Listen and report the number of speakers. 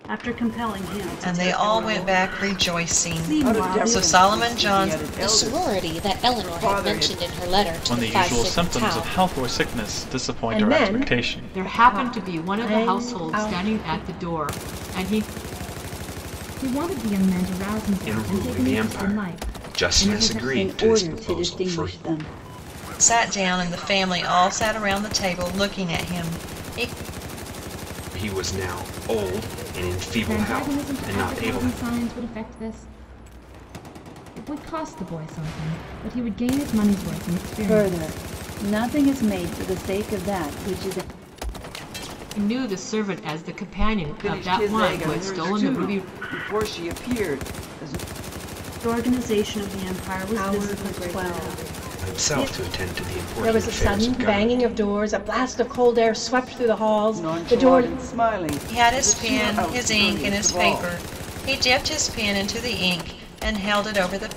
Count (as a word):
ten